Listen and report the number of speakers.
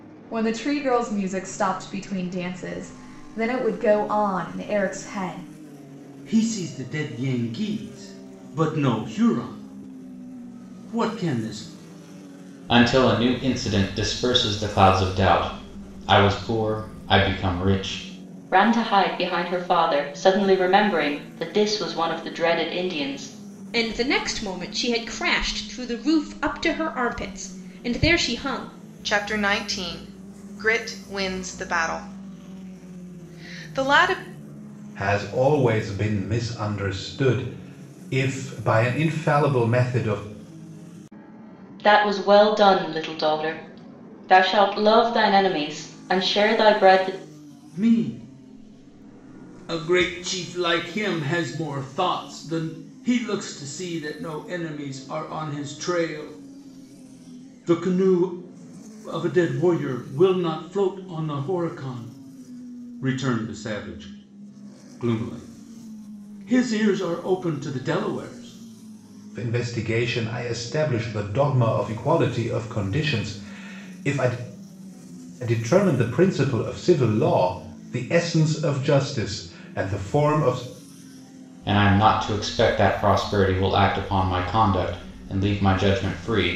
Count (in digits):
7